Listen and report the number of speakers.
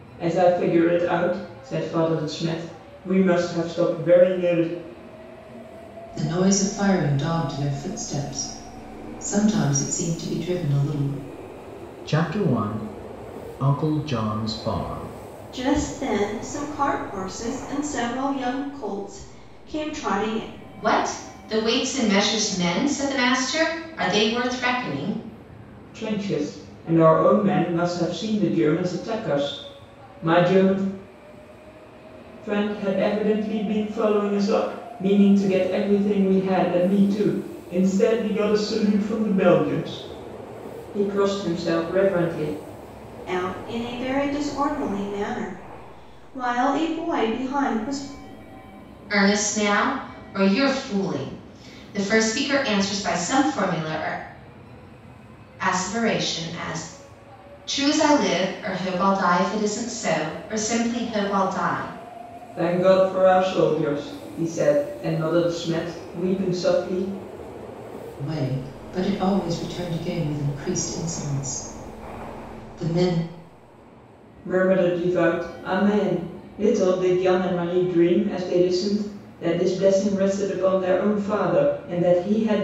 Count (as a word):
five